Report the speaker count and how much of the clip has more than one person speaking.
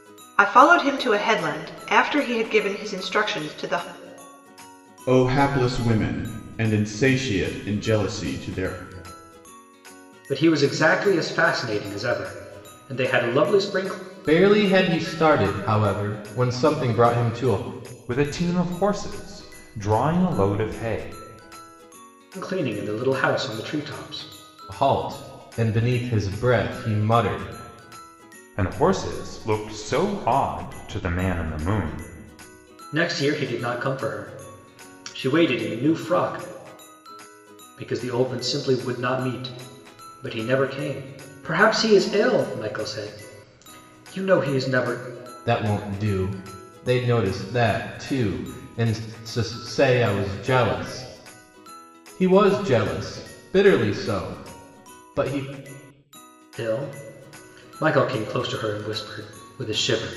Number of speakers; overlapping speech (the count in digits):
5, no overlap